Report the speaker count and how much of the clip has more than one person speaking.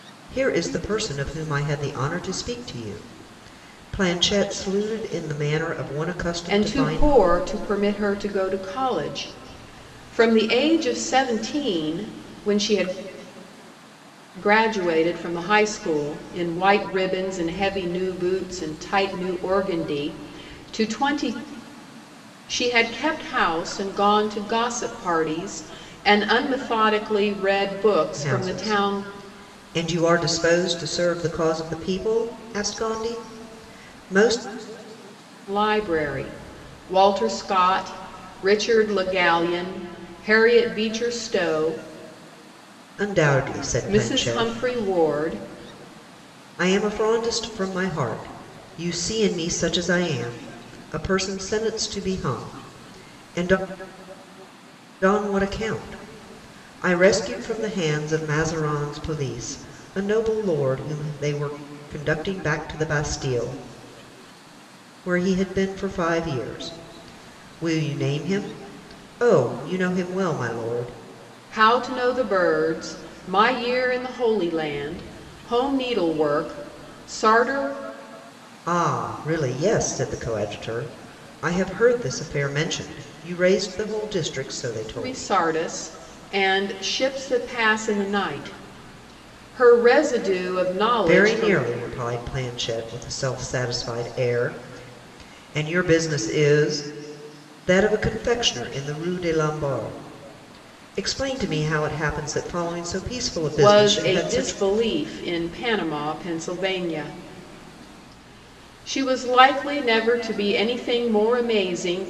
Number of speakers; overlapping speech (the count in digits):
2, about 4%